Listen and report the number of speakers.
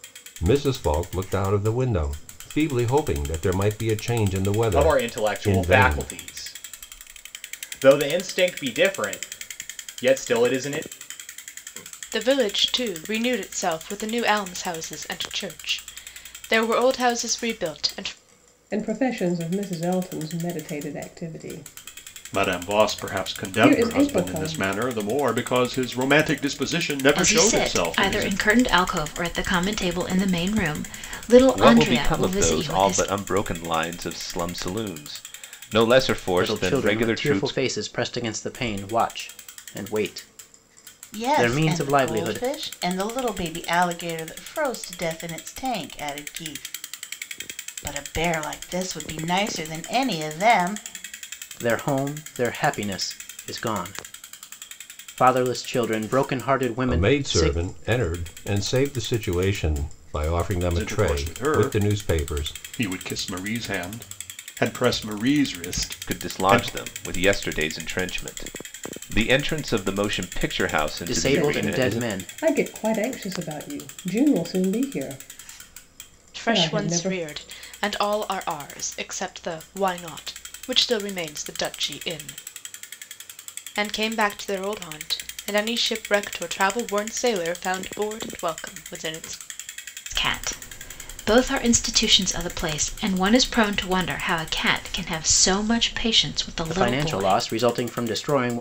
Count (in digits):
9